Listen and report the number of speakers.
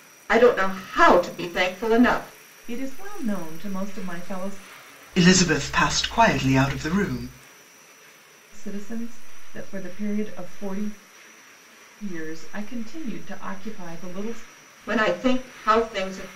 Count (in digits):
3